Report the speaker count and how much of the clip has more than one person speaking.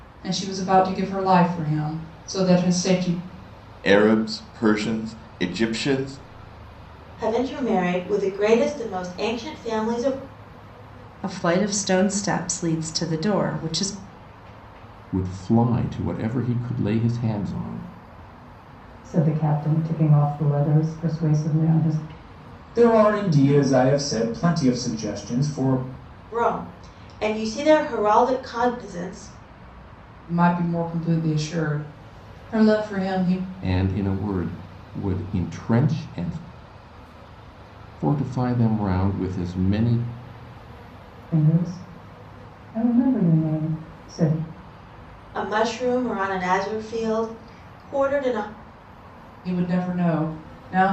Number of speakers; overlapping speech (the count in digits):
7, no overlap